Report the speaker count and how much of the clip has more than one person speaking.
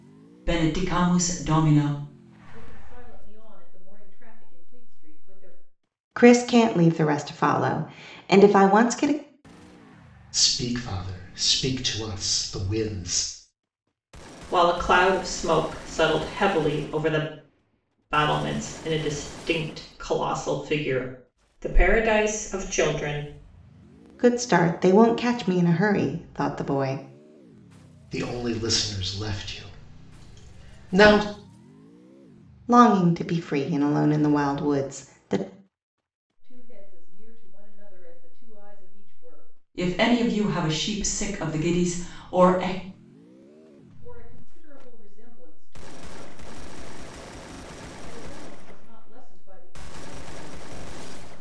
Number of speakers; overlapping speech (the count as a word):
five, no overlap